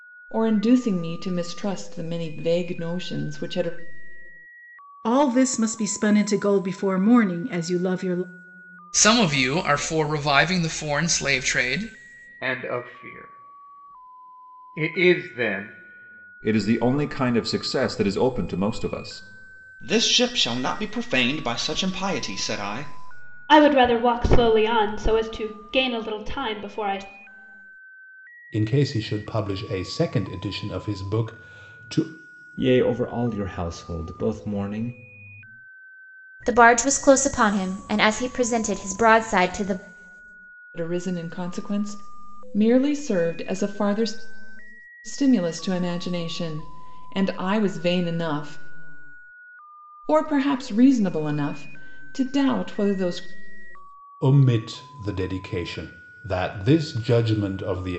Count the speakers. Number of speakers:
10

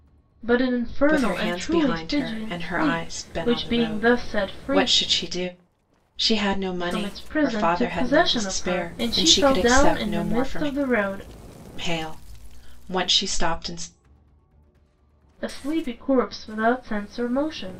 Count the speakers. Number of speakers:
2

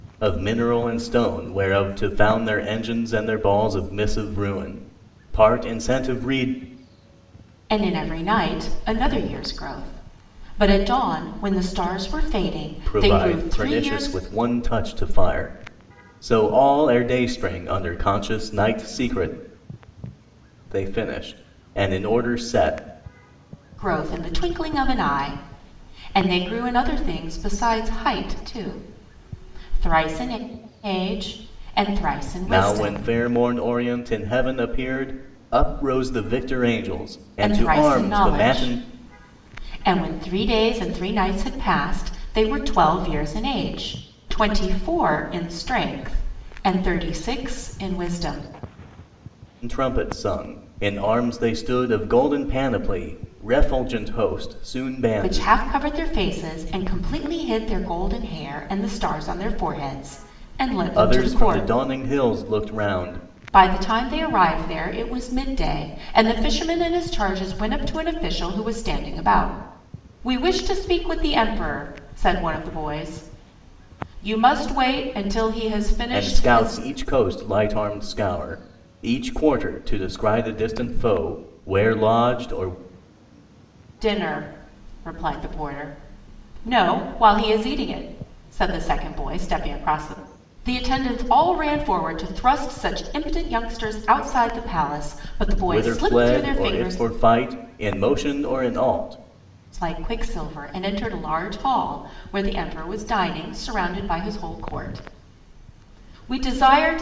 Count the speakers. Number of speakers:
2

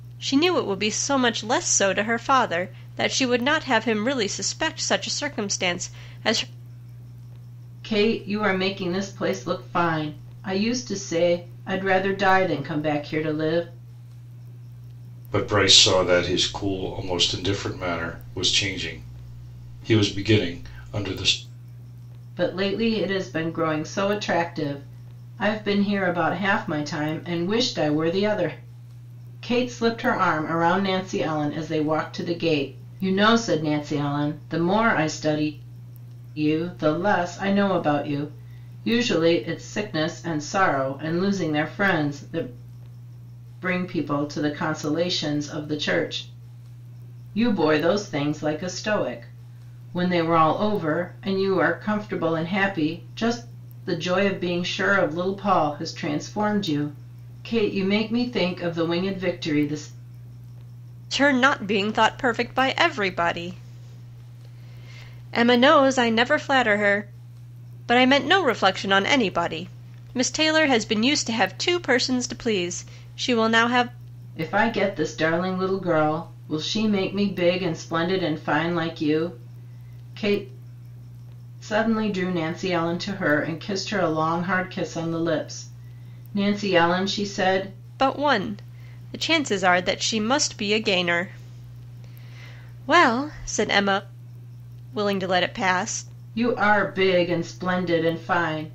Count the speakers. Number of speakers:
3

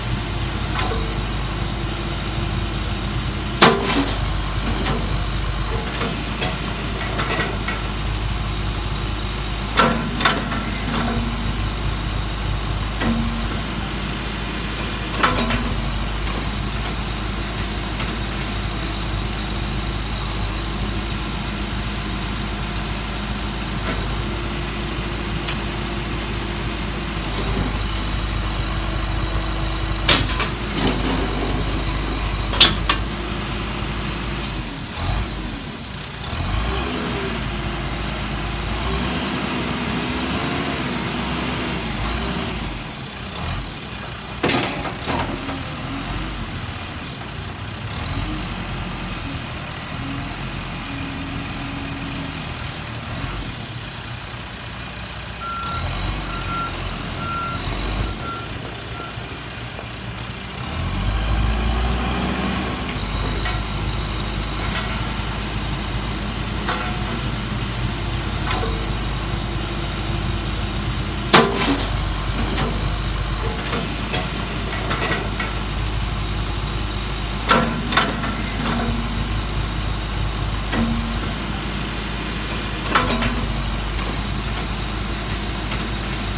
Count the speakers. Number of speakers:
0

